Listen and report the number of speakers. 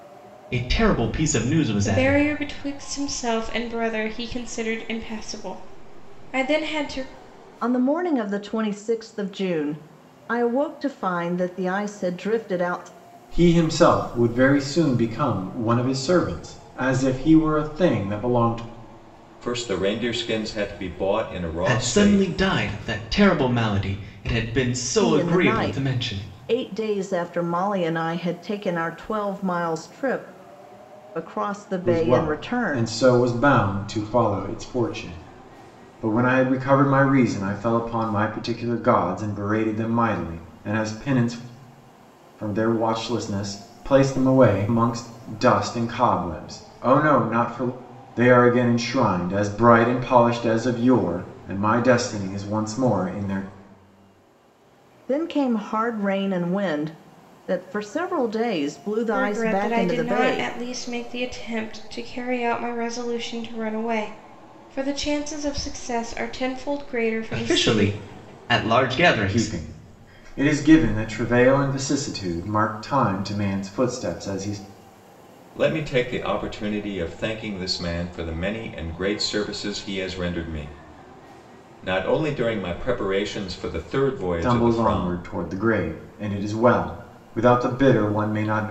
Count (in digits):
5